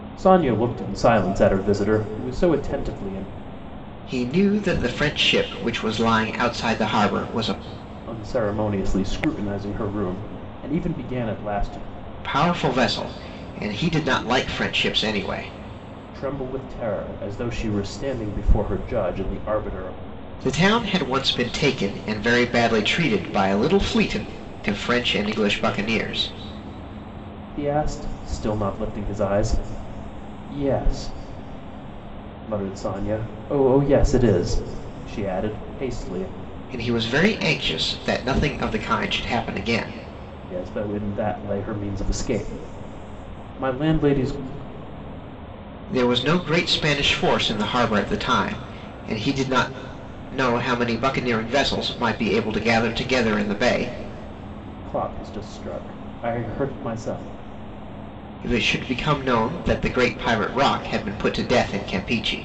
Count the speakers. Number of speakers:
2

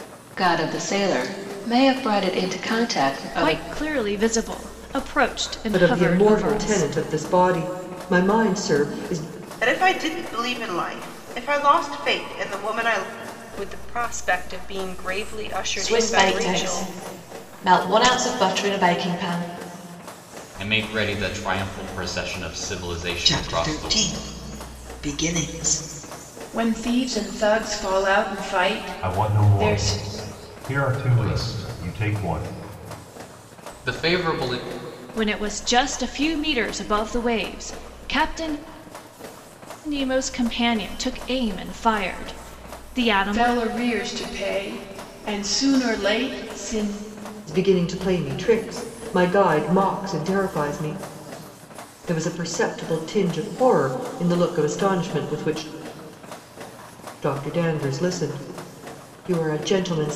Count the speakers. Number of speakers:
10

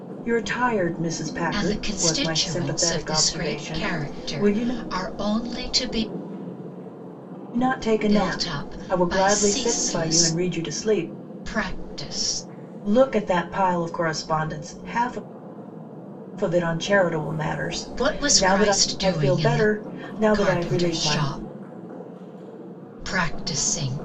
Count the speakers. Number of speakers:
2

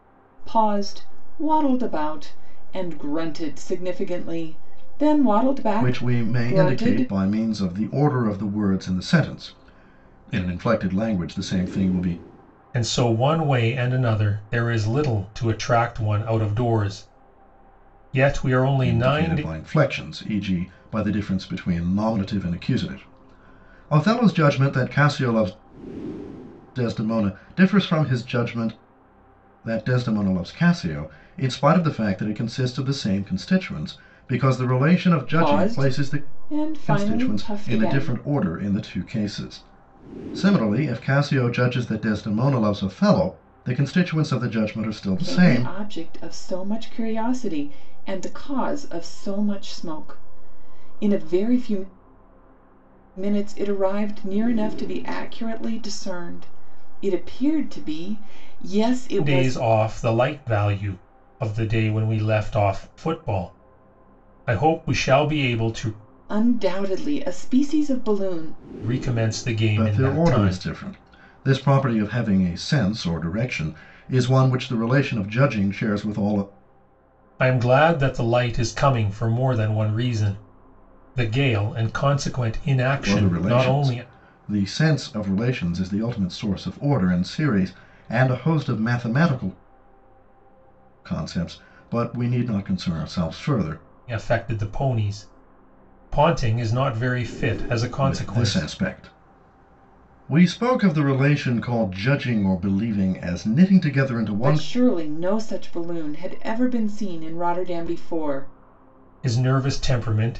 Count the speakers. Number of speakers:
3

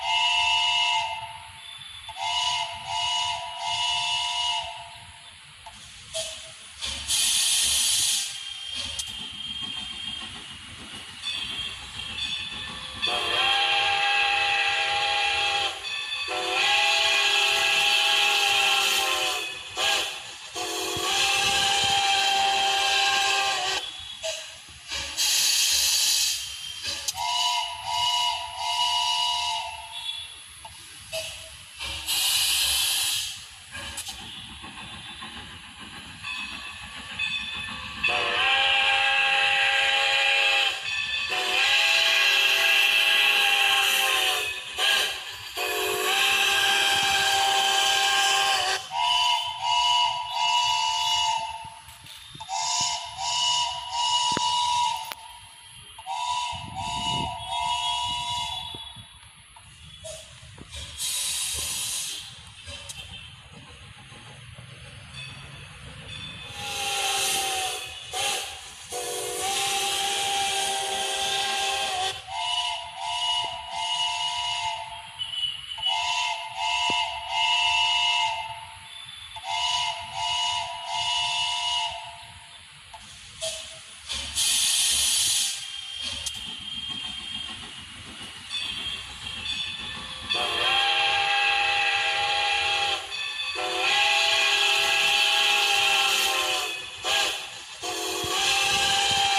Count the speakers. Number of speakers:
0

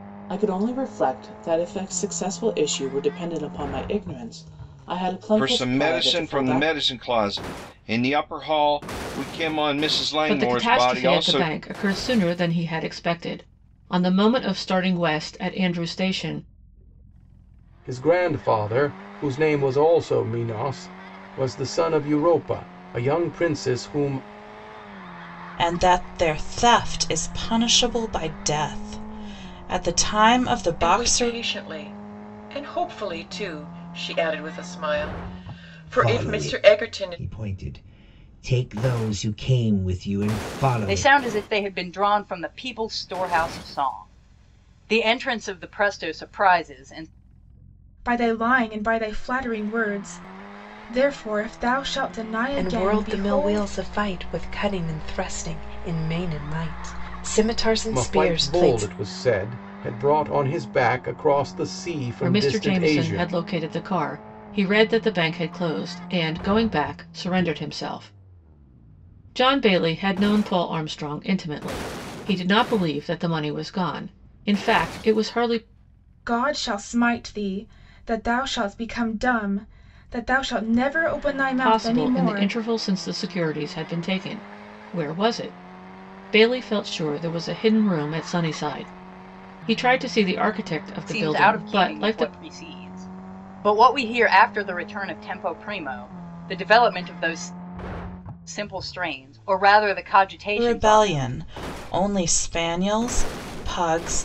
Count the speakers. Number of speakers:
10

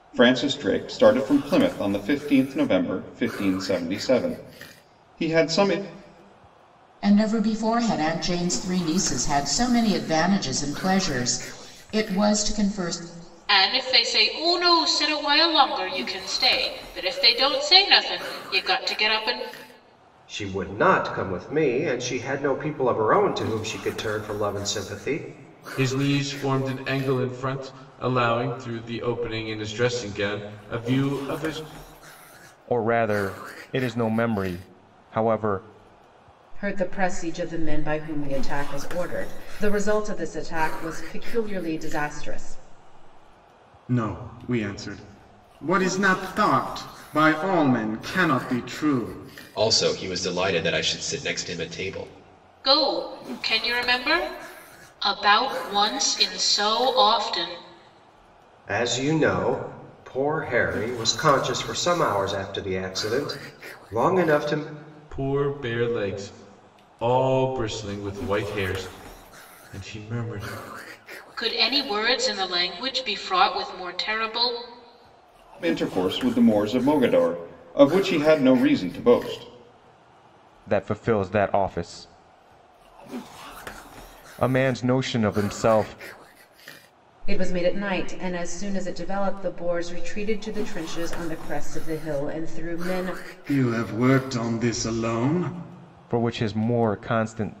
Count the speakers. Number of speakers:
9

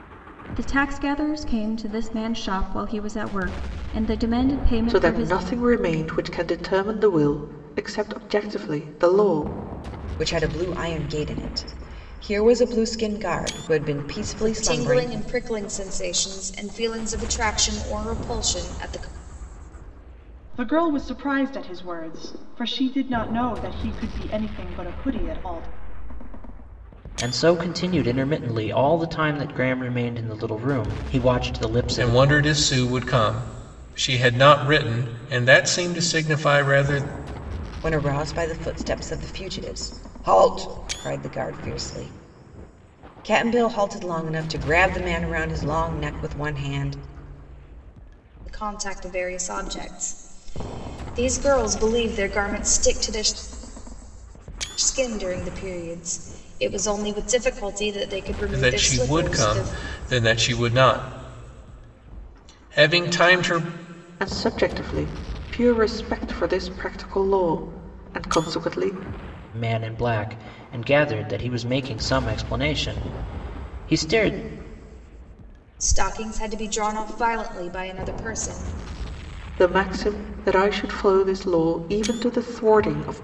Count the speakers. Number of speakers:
7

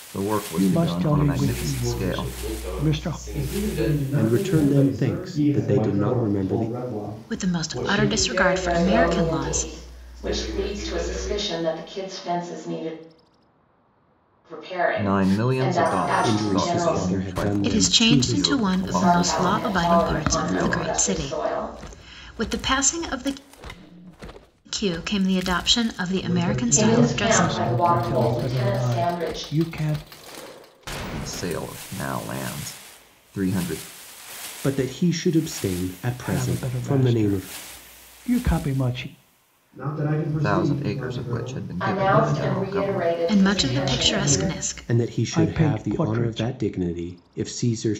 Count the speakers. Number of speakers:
8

